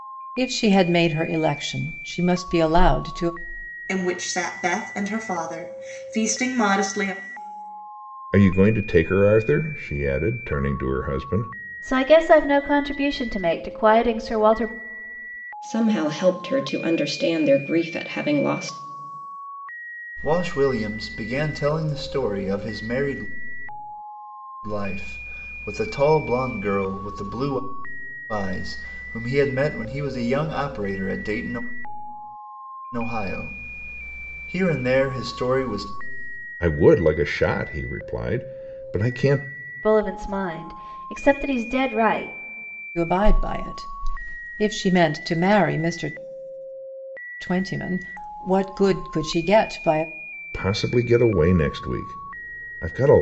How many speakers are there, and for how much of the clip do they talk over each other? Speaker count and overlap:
six, no overlap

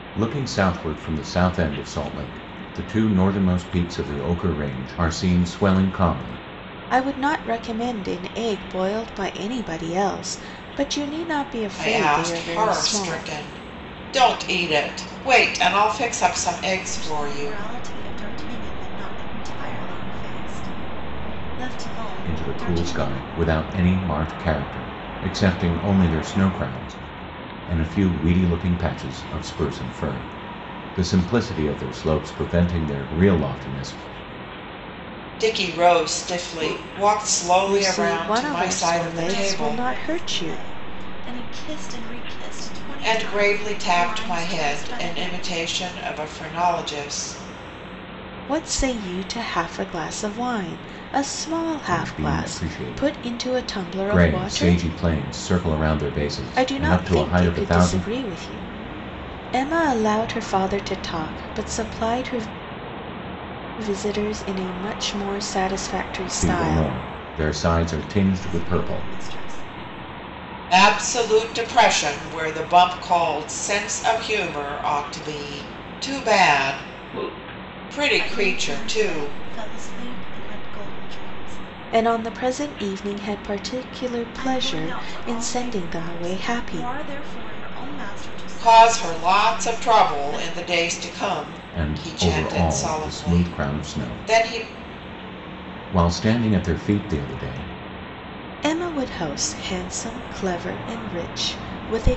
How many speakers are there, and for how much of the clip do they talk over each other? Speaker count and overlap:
four, about 23%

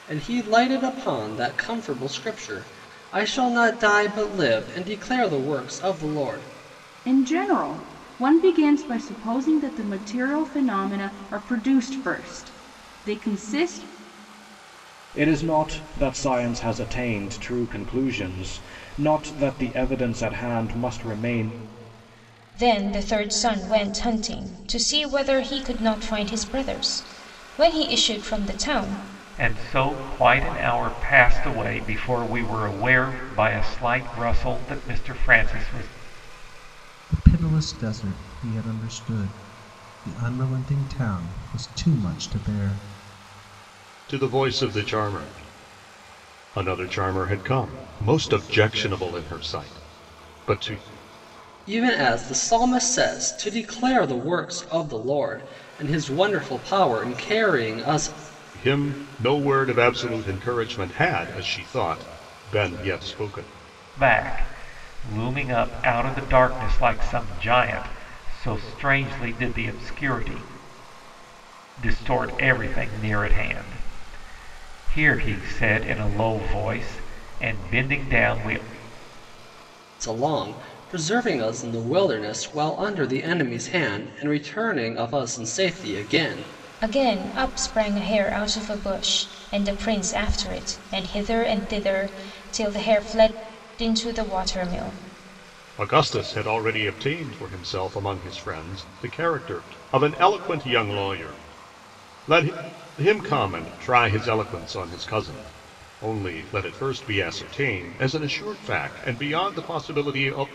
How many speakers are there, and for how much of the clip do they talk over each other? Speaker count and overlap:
seven, no overlap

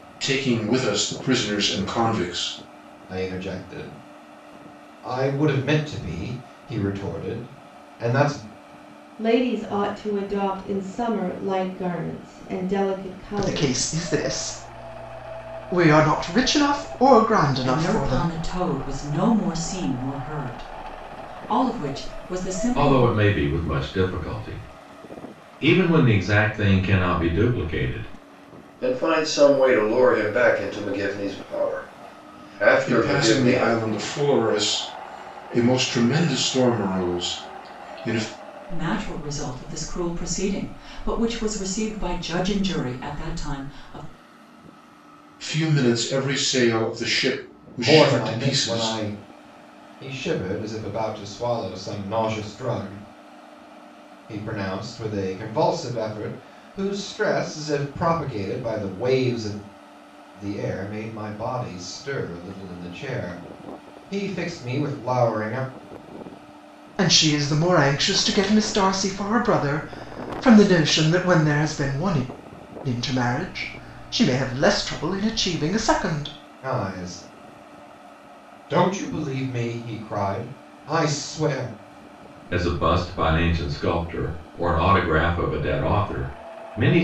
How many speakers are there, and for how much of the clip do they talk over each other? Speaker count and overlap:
seven, about 4%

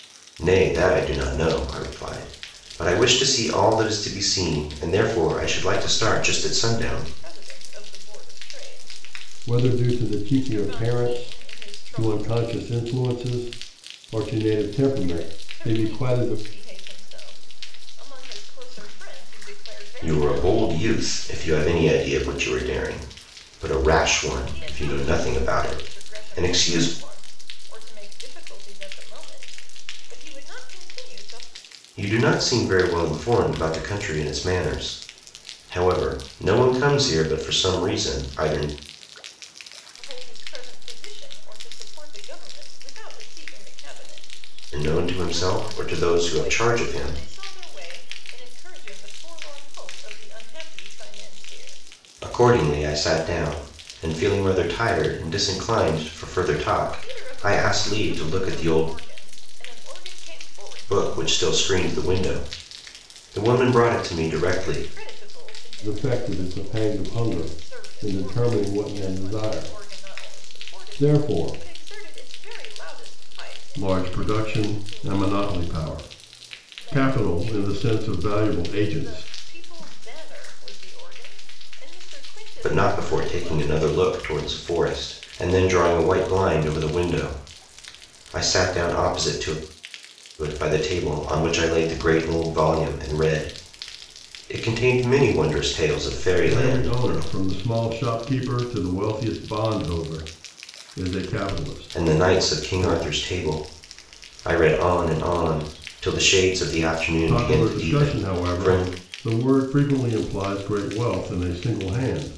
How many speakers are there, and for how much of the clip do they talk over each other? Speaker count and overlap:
three, about 29%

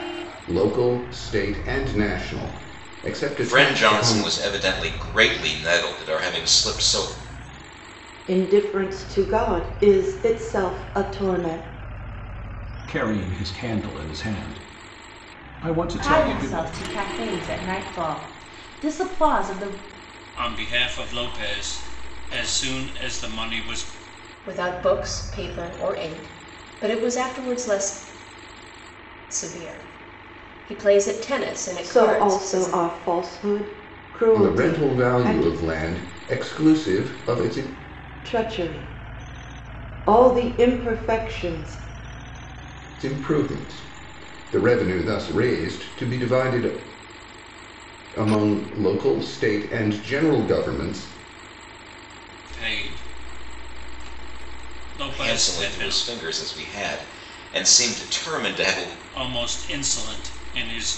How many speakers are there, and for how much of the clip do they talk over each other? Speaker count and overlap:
seven, about 7%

